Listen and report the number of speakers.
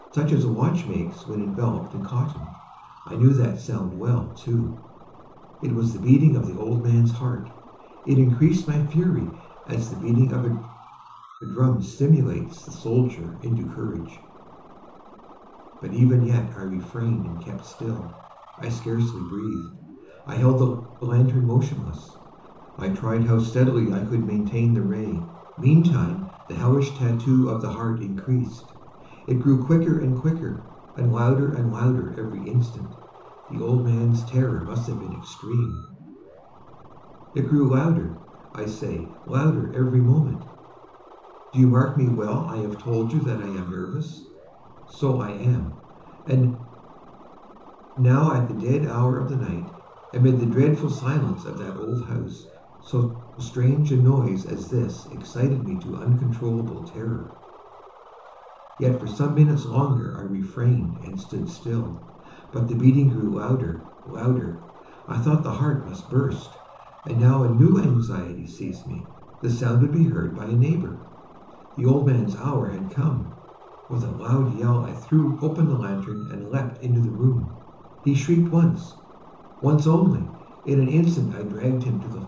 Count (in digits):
1